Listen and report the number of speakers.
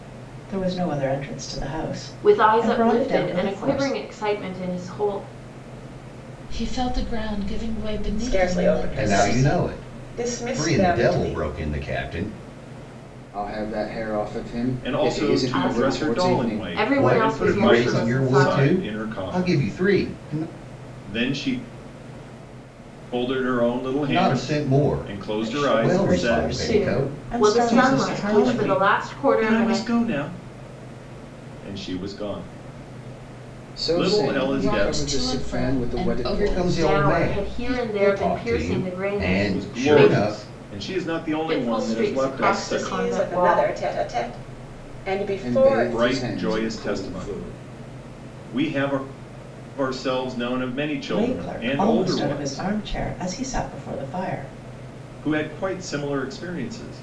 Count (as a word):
seven